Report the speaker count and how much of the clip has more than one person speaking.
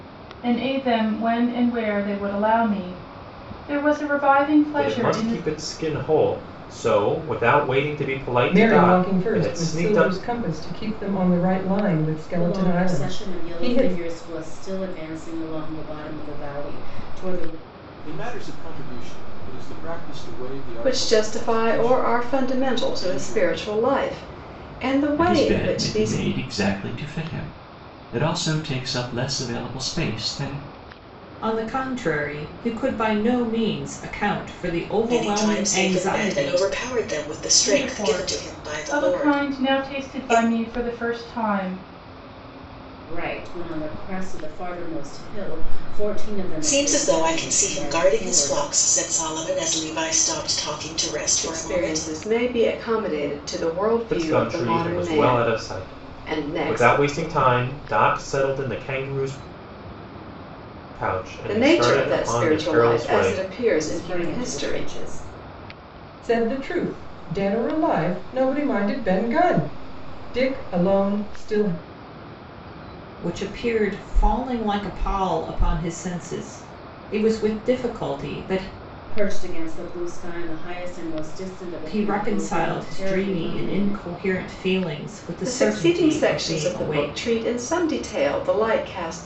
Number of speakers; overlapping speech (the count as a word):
nine, about 28%